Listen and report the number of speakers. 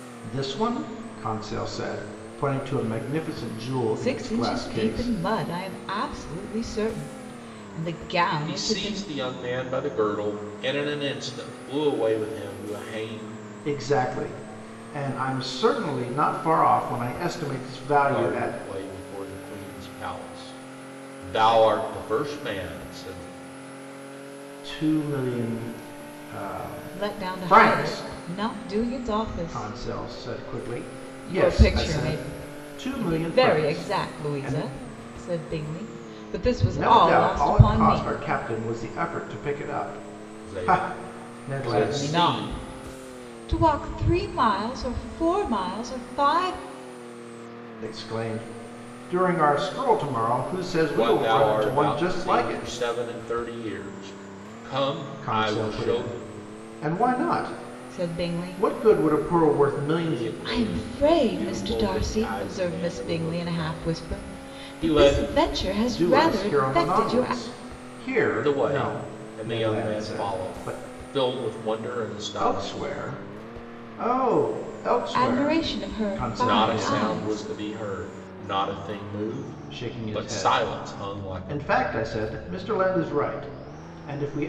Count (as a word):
three